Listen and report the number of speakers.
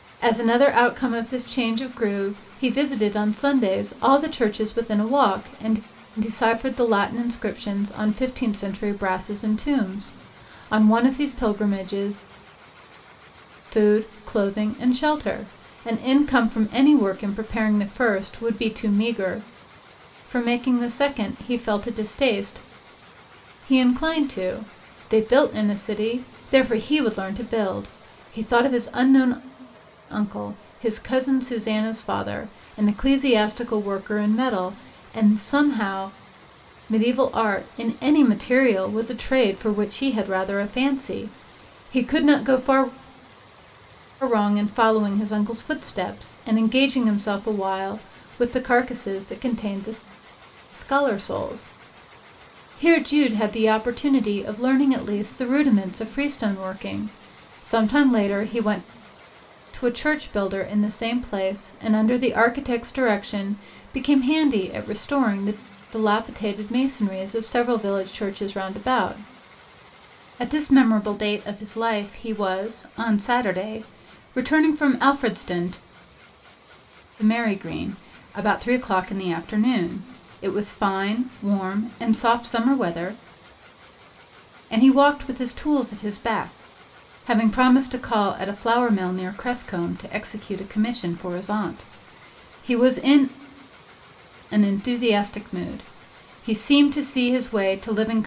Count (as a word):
one